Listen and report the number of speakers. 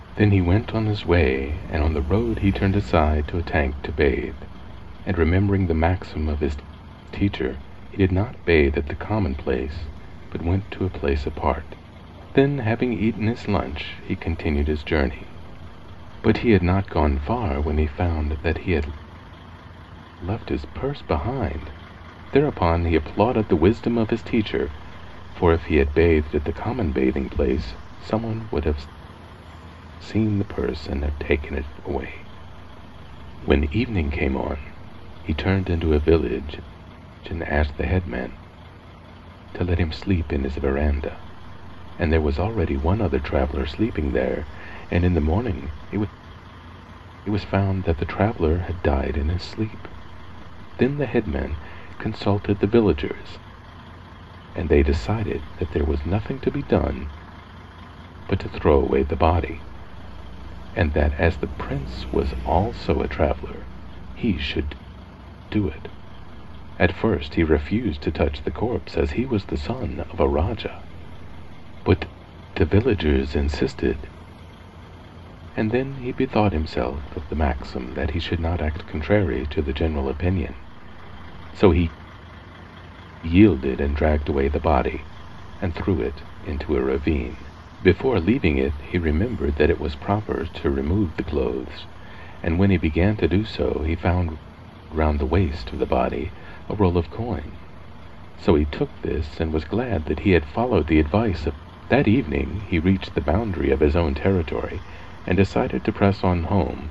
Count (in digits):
1